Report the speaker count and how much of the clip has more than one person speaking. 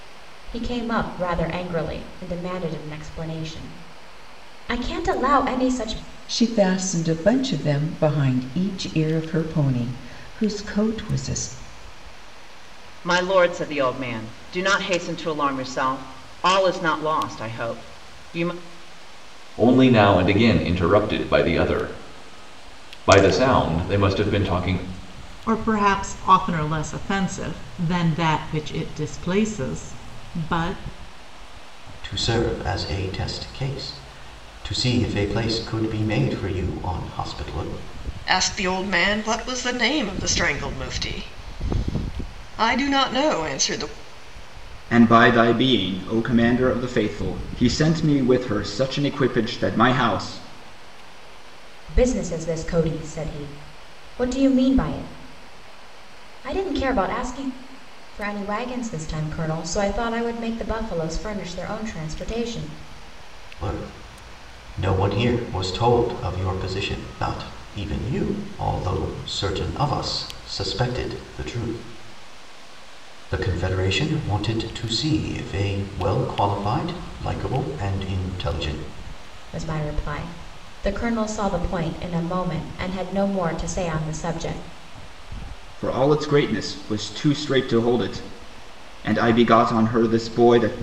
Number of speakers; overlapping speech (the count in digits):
8, no overlap